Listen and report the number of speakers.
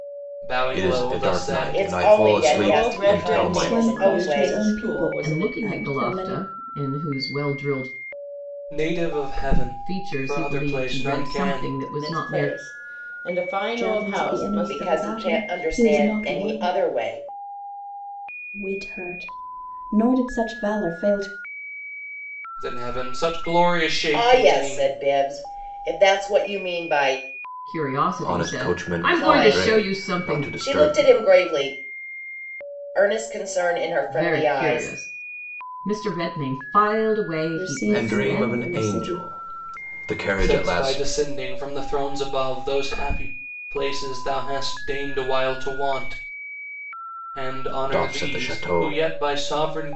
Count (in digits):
6